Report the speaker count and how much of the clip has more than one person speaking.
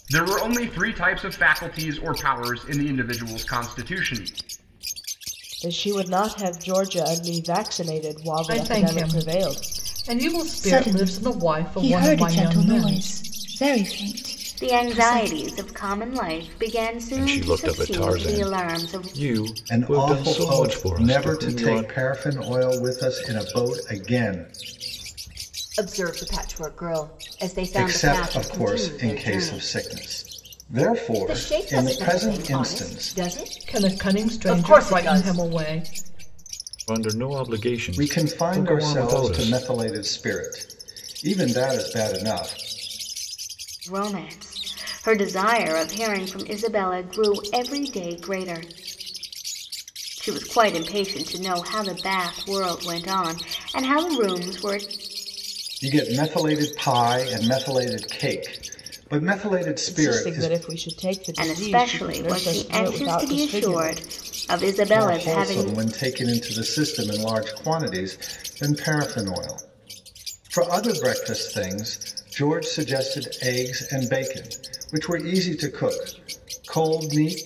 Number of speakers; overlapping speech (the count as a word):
eight, about 26%